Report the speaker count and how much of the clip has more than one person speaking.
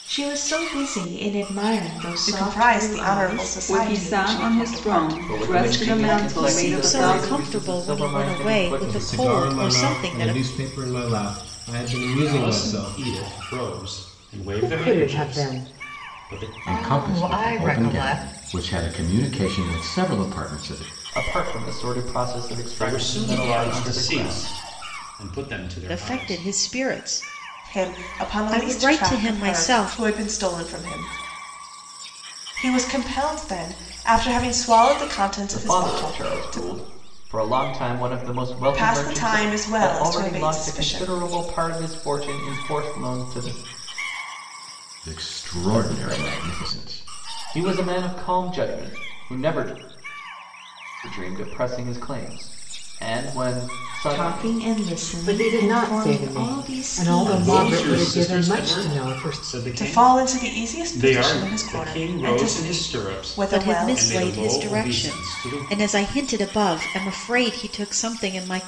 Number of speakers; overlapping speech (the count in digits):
9, about 48%